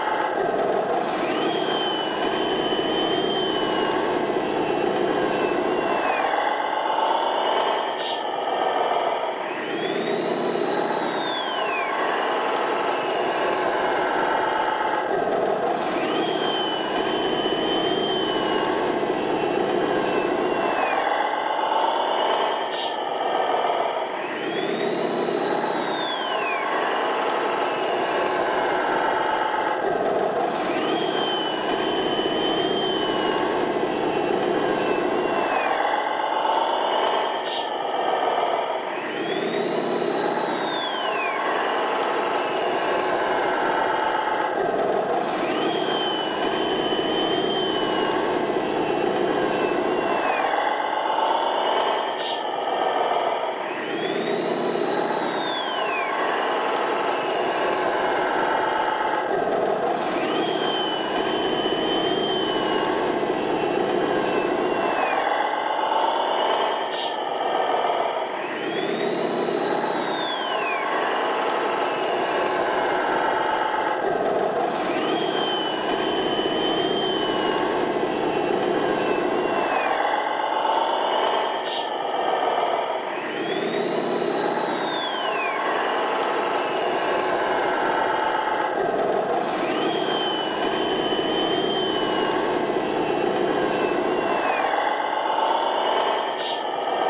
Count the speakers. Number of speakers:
0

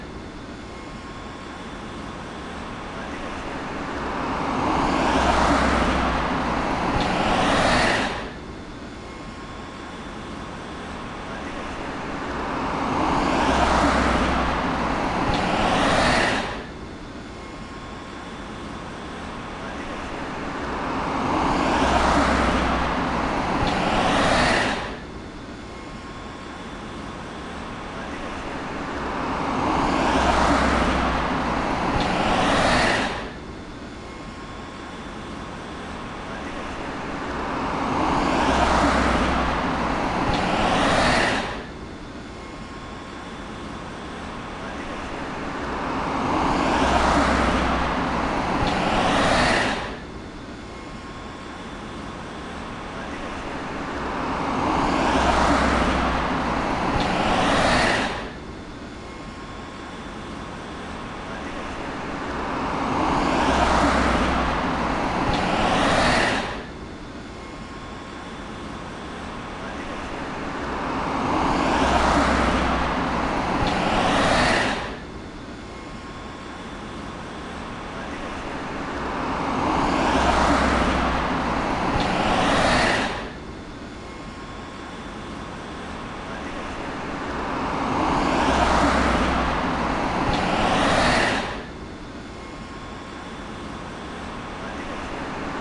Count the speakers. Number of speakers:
0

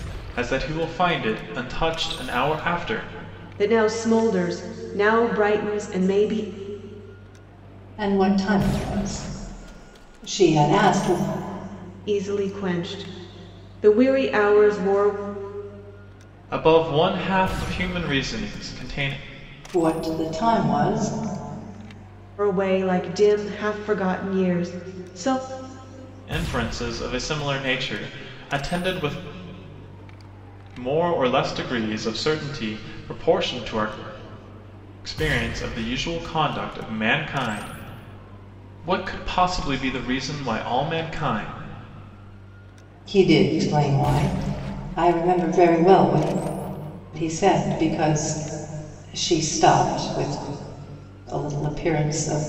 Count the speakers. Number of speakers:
3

